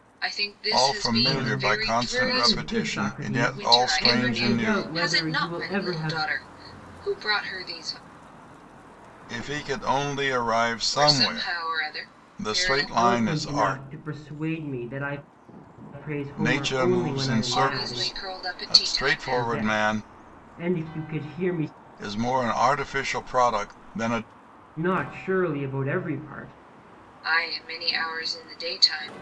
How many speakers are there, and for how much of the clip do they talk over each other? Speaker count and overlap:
three, about 39%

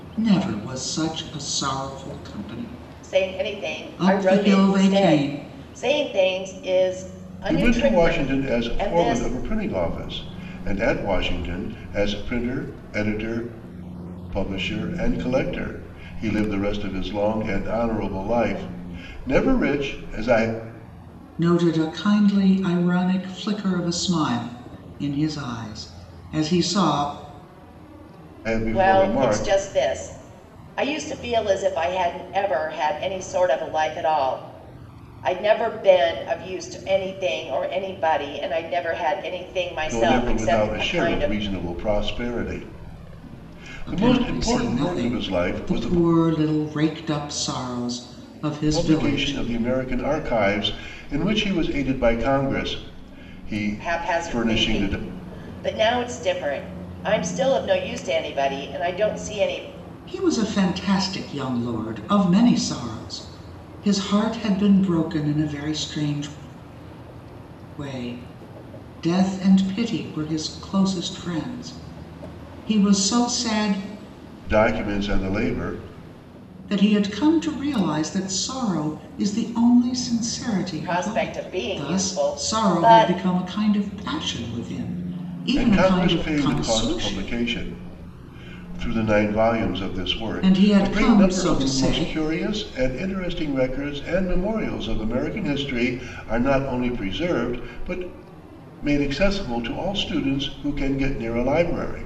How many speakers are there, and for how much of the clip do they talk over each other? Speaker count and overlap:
three, about 17%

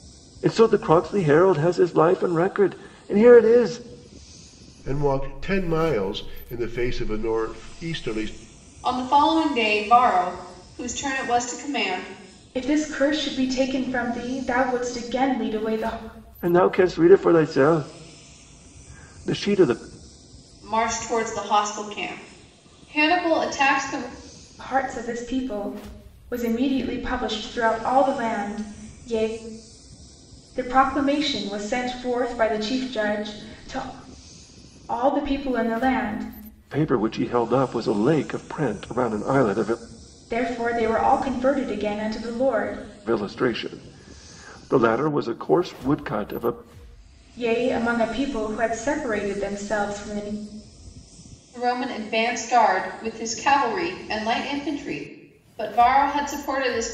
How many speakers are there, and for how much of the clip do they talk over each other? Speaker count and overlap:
four, no overlap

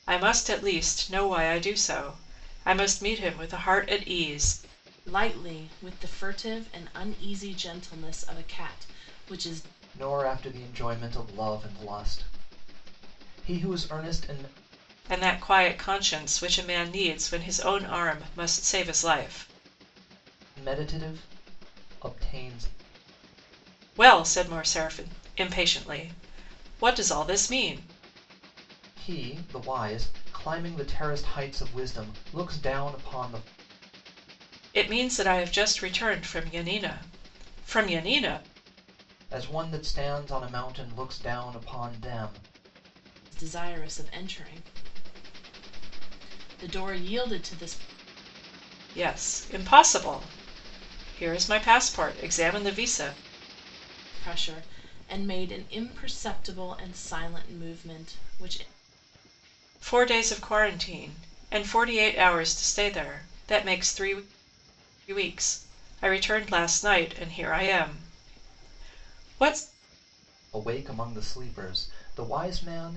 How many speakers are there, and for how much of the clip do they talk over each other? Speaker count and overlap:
three, no overlap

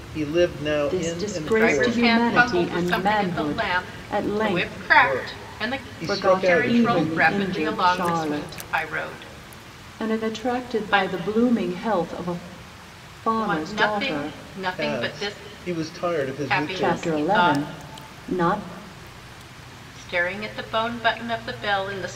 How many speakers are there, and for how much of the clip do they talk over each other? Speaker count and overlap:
three, about 59%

